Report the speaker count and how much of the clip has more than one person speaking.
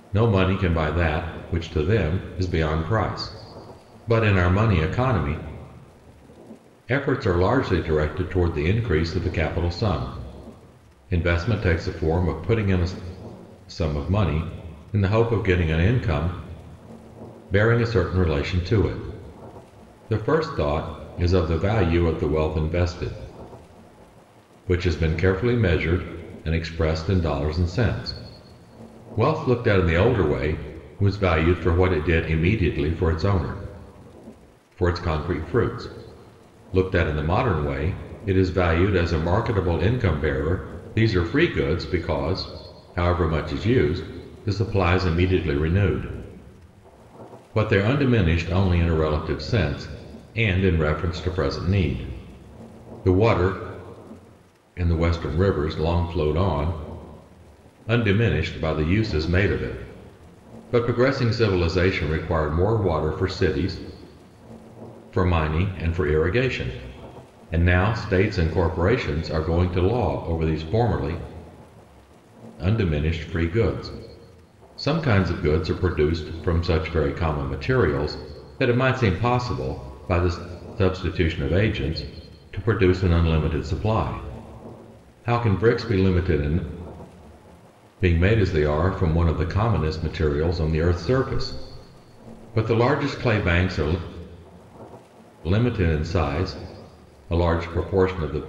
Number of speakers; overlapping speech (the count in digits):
1, no overlap